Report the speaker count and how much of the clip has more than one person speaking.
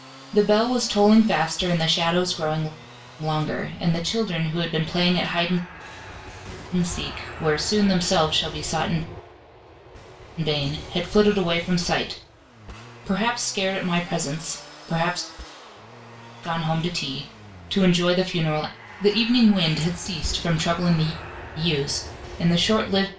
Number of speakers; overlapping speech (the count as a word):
one, no overlap